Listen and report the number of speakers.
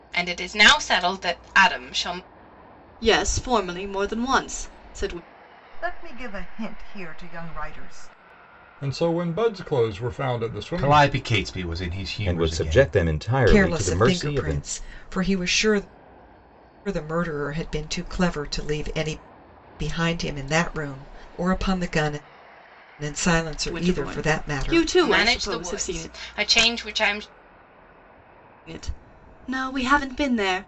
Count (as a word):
seven